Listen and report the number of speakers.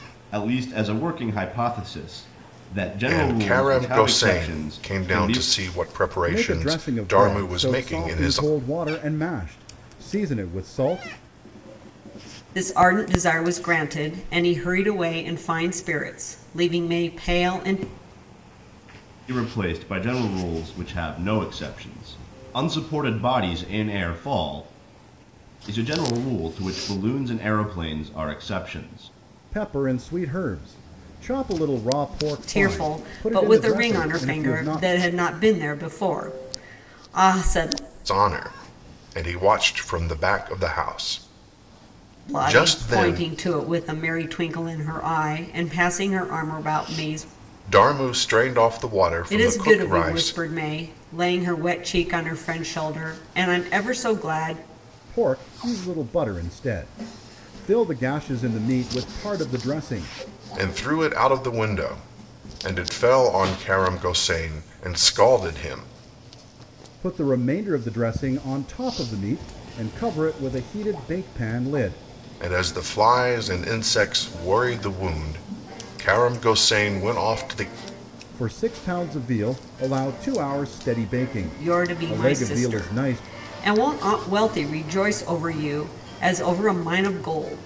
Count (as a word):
four